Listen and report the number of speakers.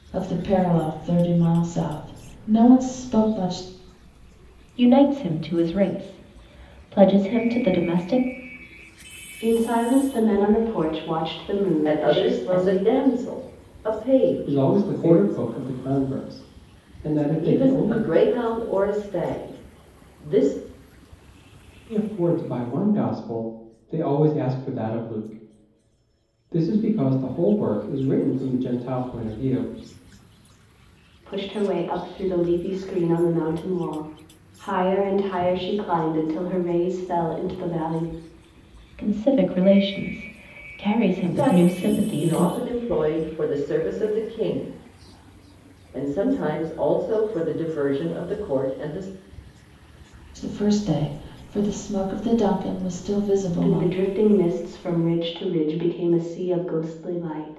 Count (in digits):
5